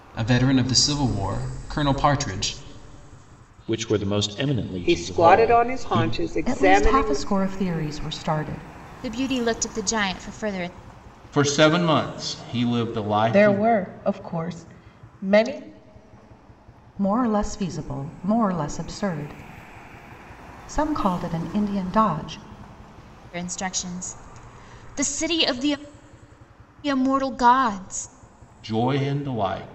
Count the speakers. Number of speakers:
seven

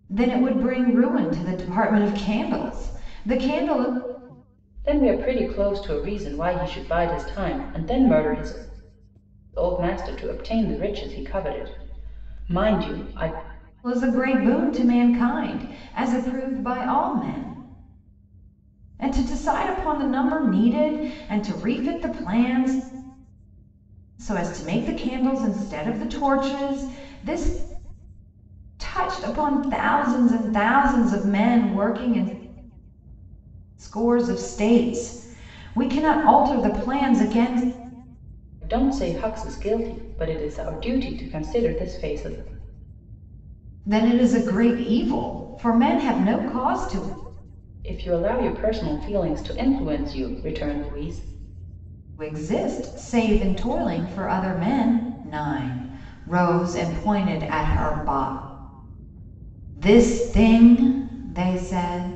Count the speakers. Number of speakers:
two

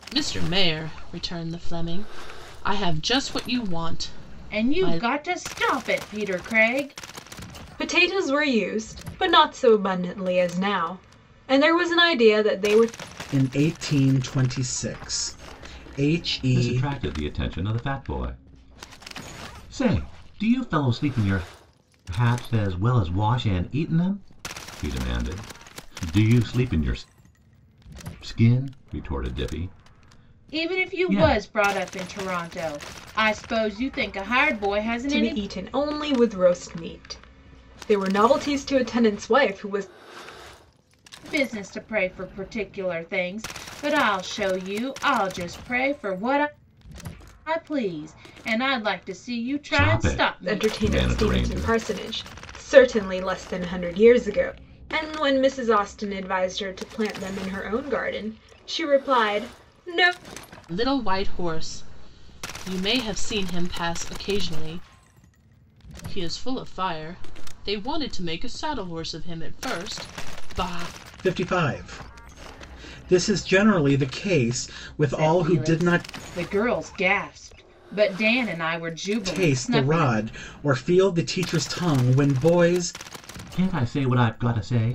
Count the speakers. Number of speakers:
five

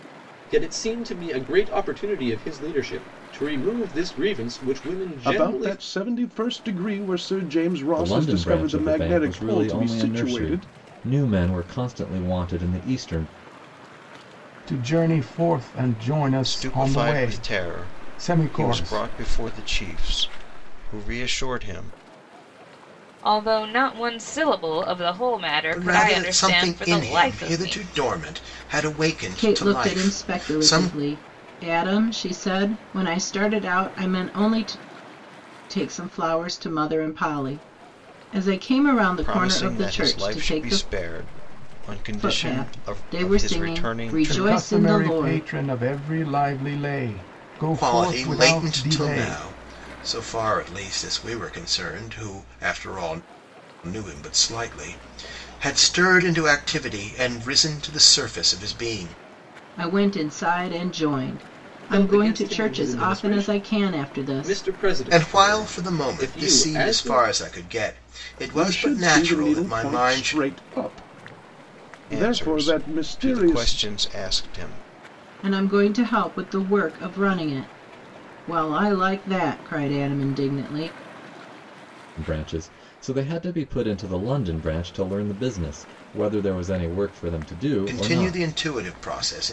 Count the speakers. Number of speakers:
eight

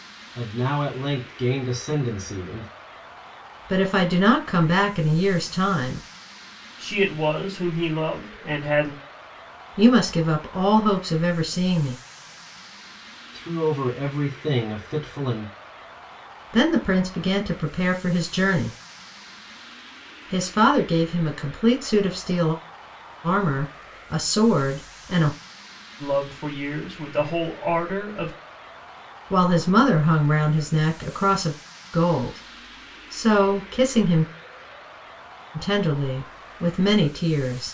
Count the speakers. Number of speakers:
three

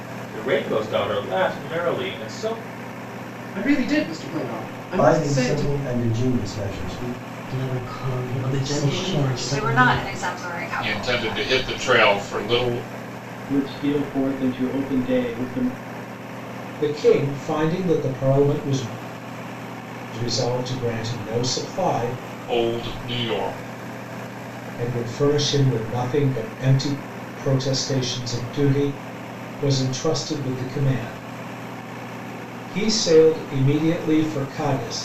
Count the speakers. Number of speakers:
nine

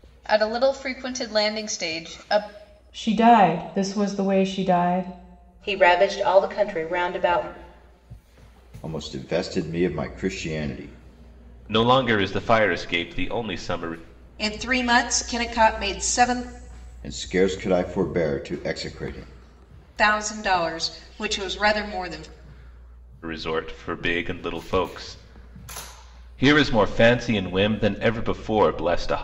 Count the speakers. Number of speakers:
six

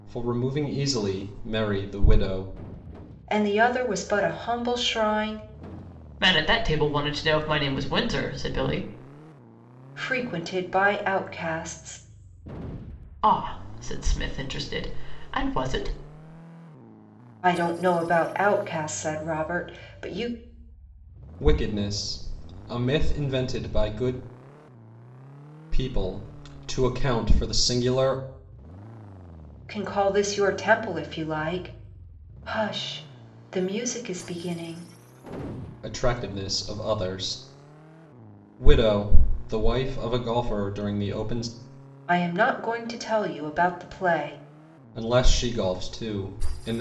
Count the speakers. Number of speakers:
three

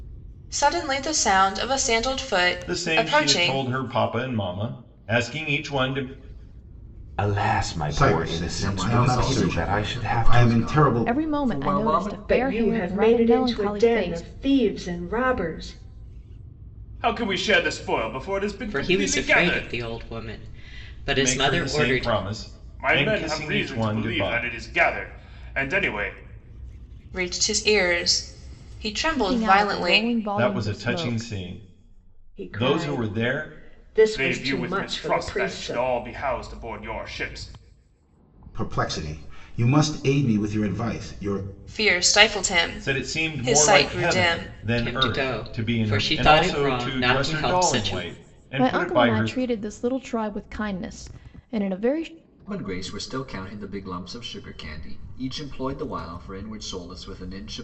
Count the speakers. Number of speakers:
nine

